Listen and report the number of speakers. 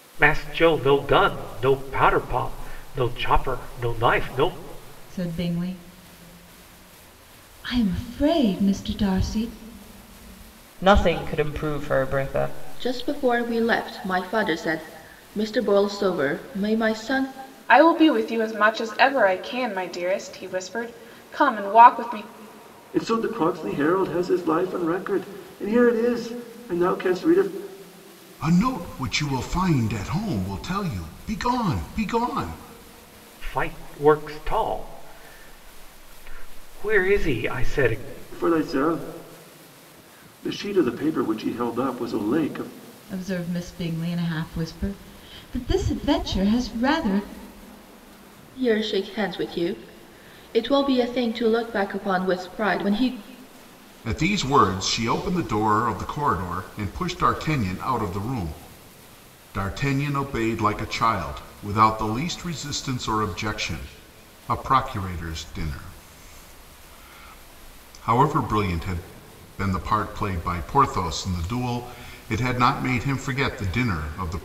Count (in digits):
7